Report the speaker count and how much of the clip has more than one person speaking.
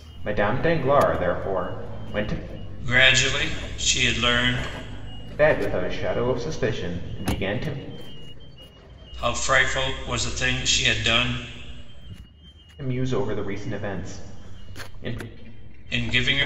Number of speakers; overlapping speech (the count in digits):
2, no overlap